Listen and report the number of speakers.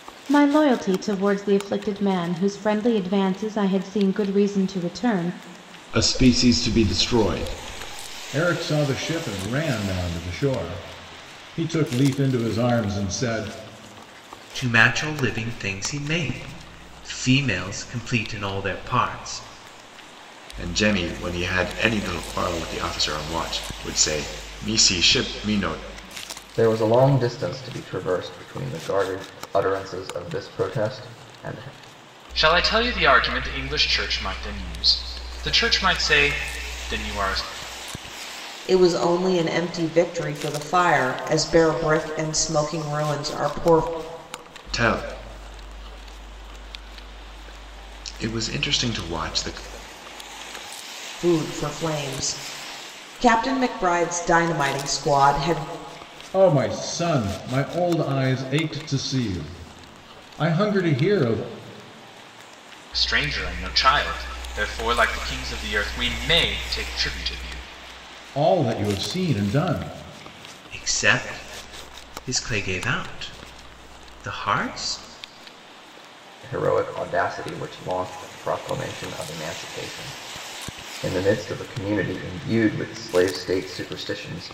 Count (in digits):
8